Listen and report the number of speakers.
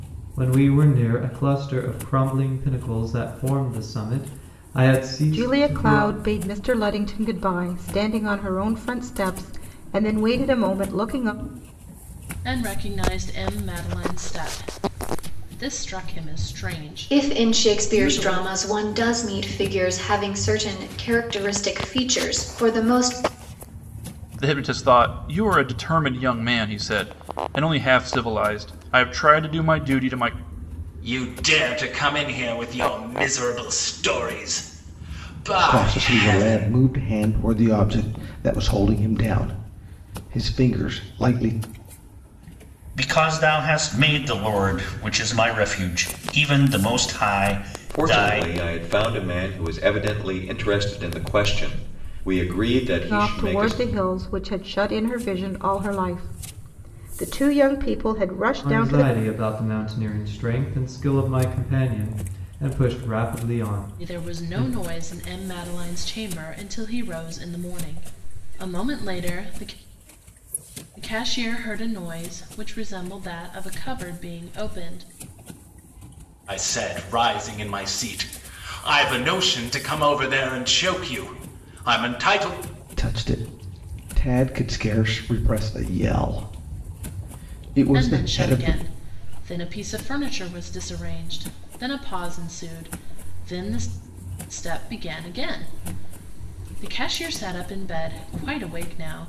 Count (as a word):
nine